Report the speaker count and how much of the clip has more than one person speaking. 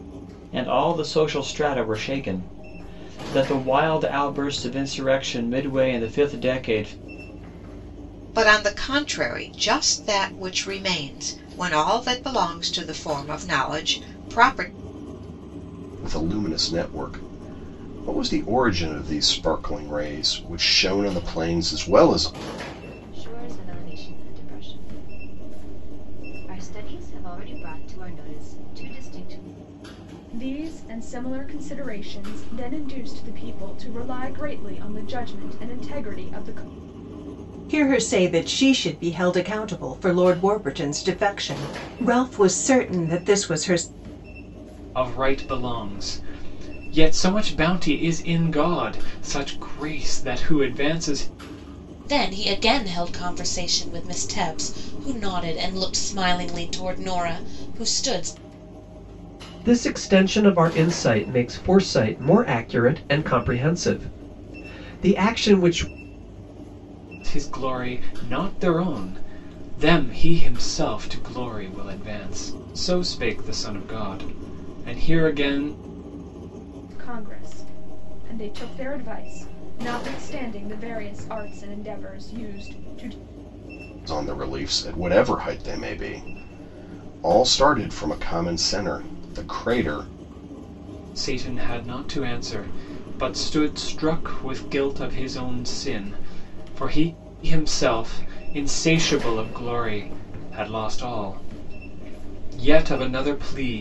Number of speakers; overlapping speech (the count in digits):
9, no overlap